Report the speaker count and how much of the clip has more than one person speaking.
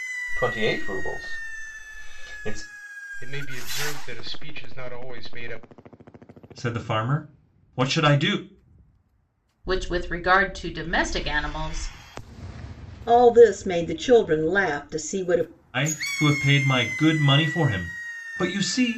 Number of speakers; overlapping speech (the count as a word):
five, no overlap